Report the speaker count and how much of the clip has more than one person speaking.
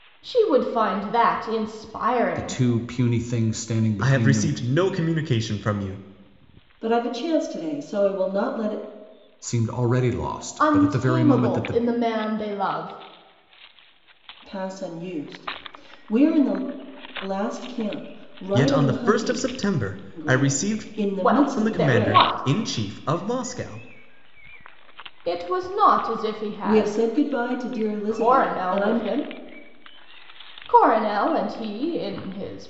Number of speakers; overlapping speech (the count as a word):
four, about 20%